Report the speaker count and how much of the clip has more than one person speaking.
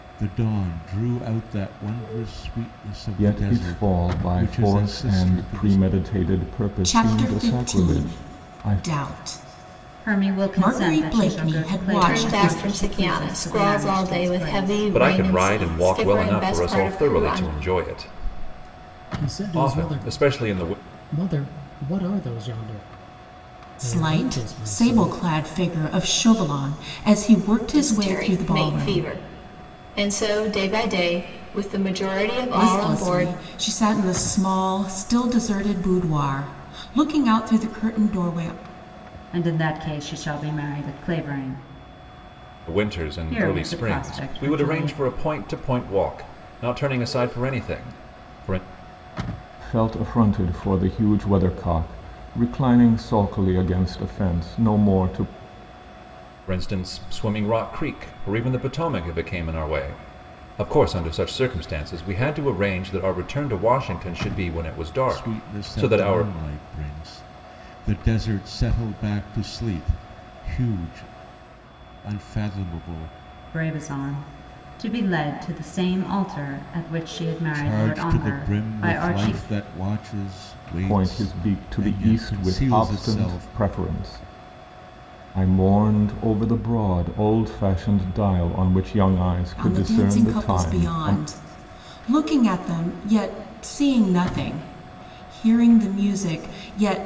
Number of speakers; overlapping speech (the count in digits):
7, about 28%